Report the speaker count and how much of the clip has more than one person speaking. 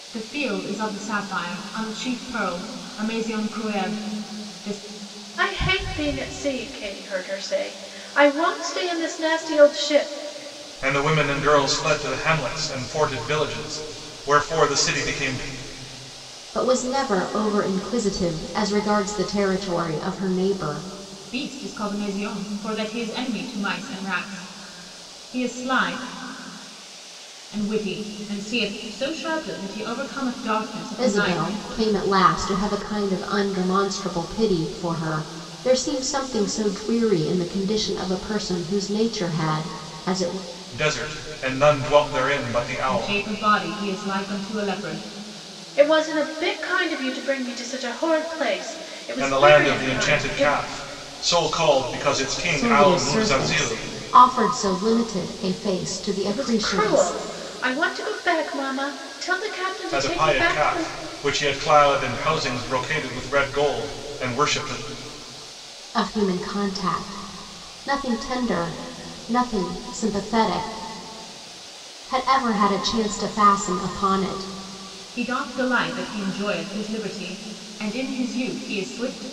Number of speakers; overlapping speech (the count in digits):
4, about 7%